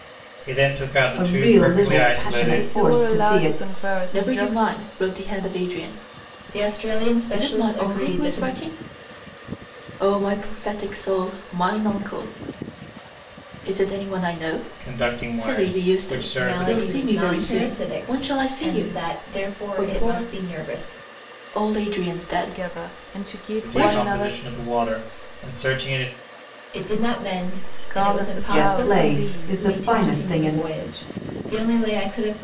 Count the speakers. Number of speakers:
6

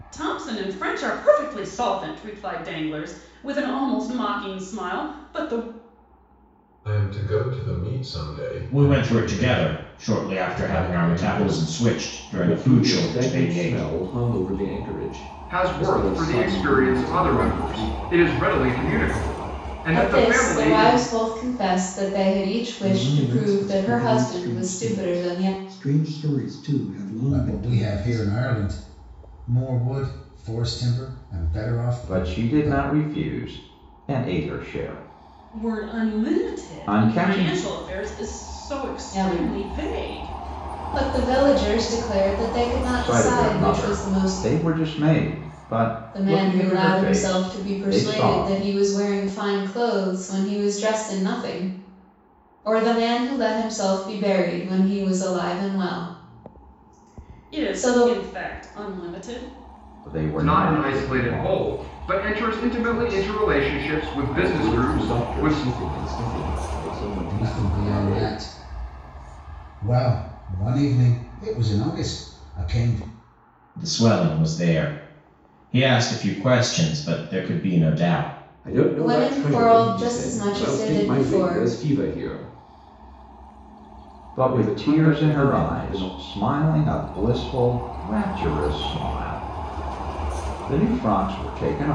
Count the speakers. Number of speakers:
9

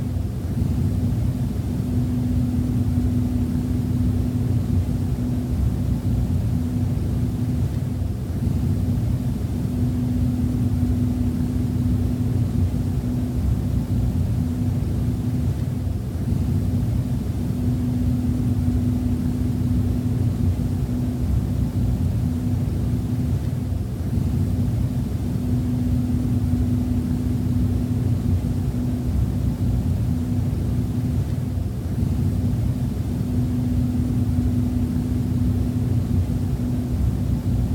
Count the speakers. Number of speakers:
0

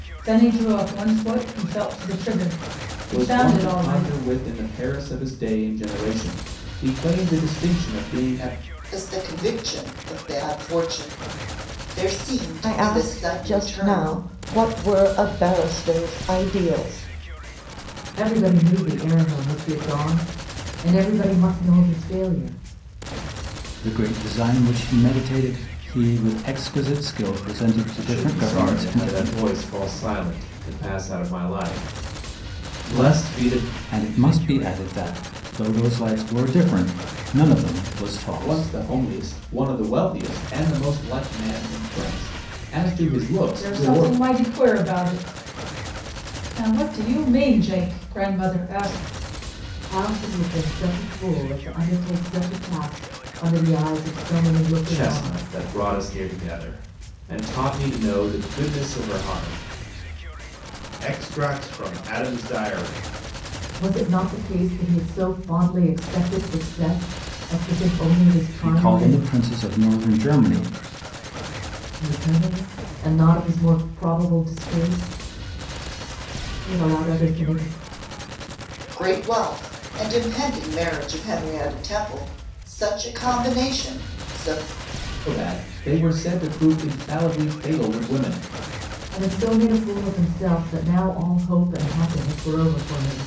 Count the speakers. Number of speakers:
7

